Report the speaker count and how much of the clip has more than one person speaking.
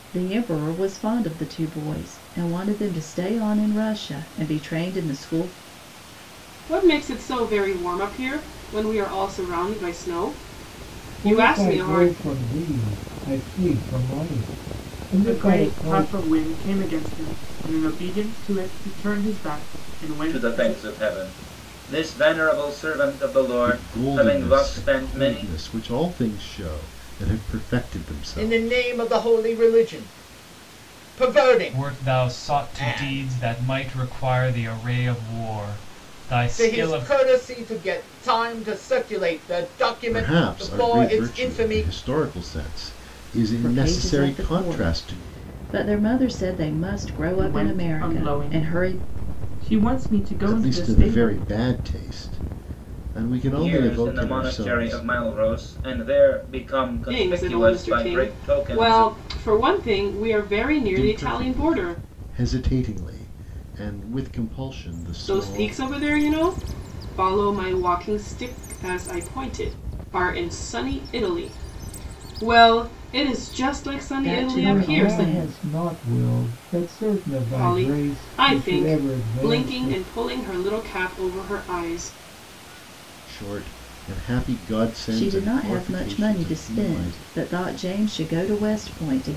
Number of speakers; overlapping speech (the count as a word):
eight, about 28%